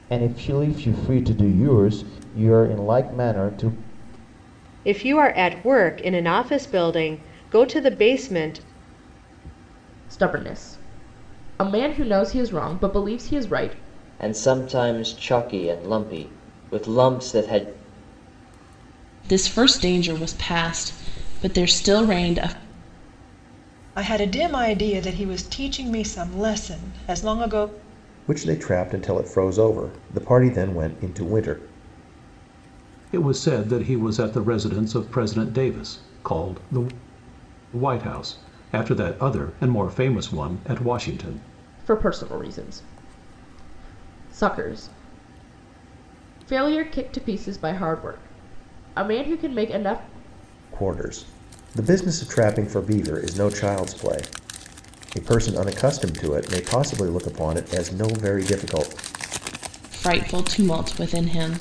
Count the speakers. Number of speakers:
8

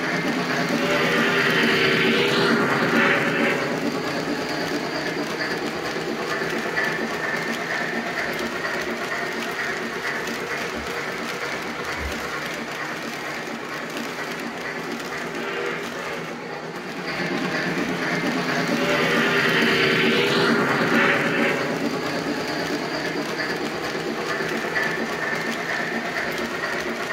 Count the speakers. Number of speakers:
0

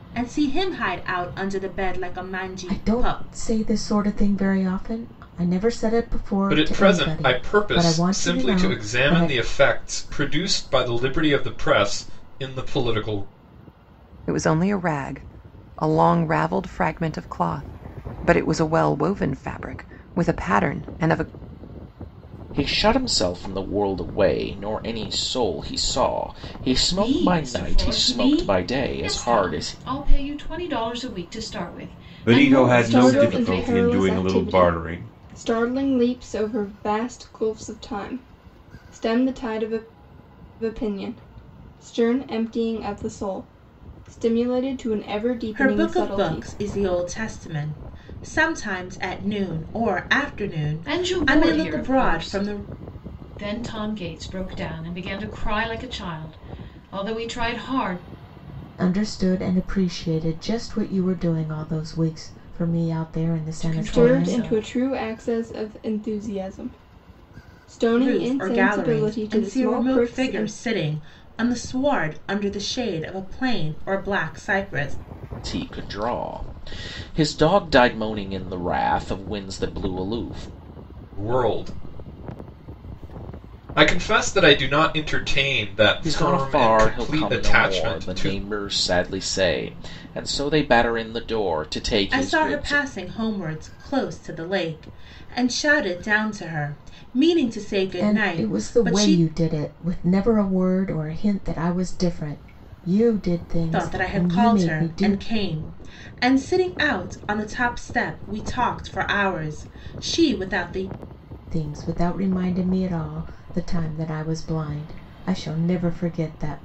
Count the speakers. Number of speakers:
8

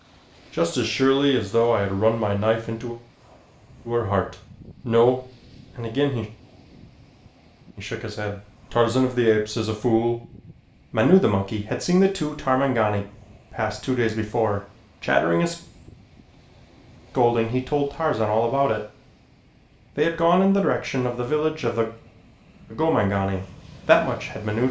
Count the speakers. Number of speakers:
1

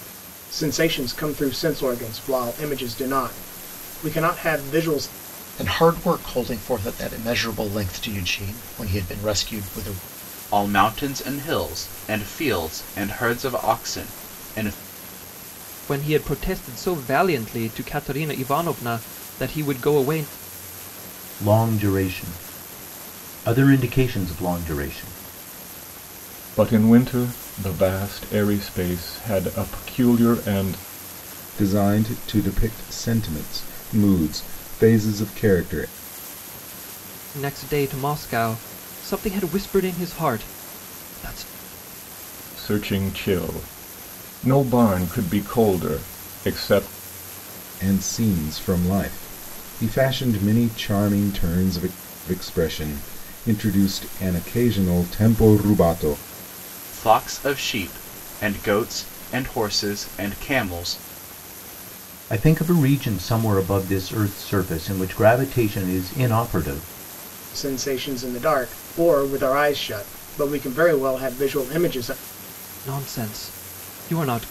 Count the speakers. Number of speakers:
7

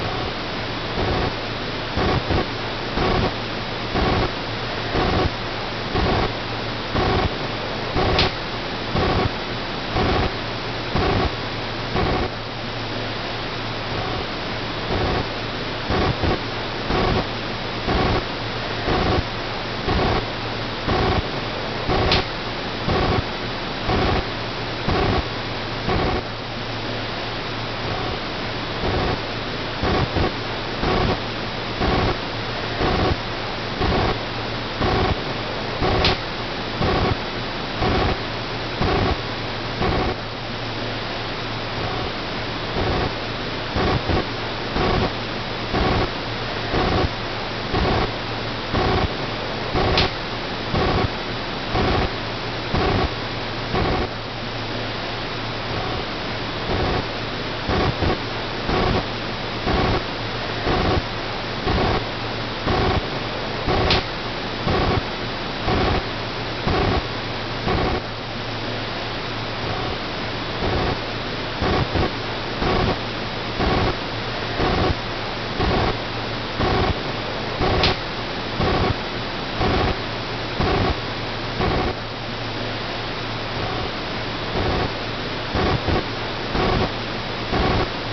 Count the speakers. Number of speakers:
0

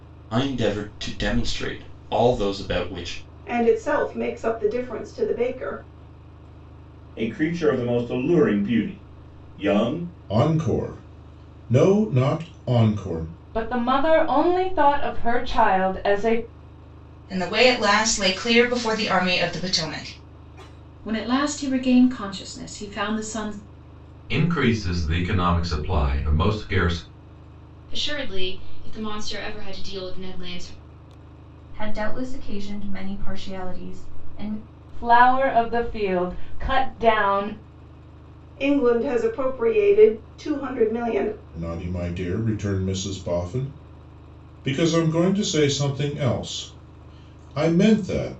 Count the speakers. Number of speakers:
10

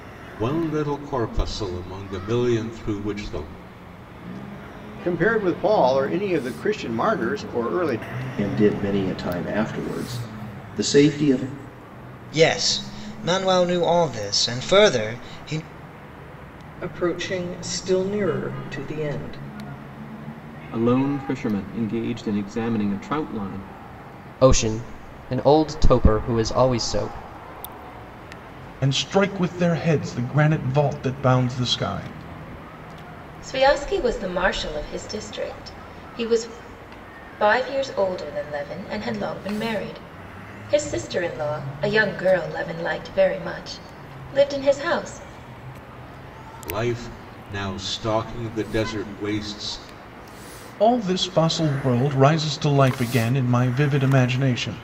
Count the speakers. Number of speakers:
9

